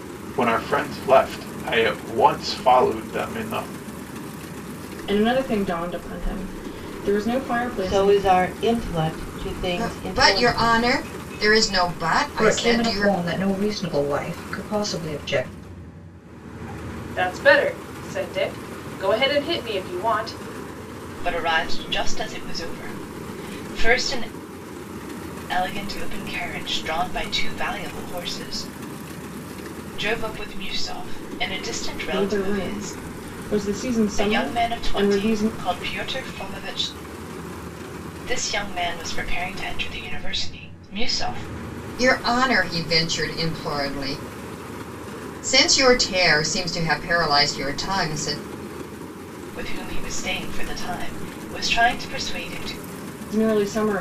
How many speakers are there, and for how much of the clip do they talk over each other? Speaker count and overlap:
seven, about 8%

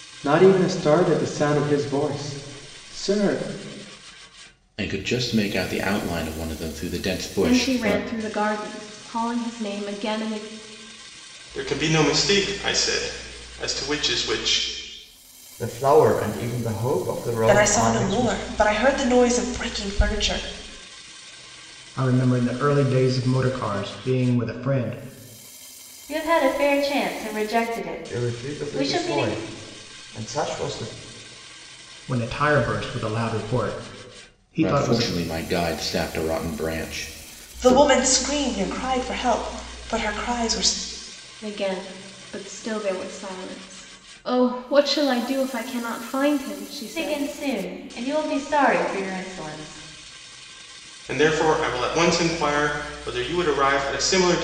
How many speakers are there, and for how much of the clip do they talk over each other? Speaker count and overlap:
eight, about 7%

